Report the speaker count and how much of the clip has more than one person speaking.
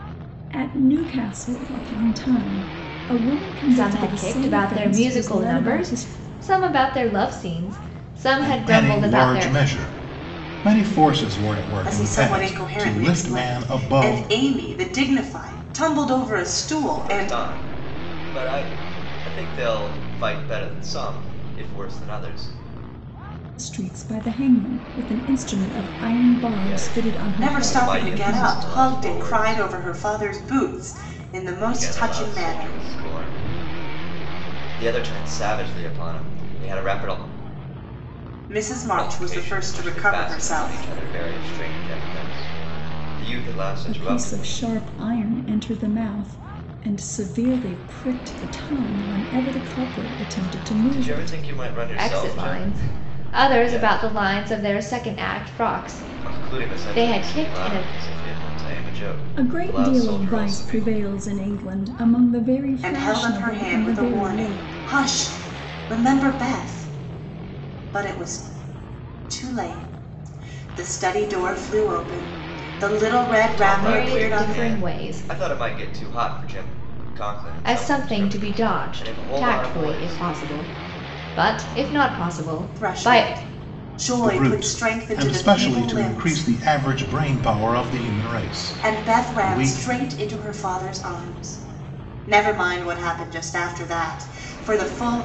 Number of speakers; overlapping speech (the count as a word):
five, about 31%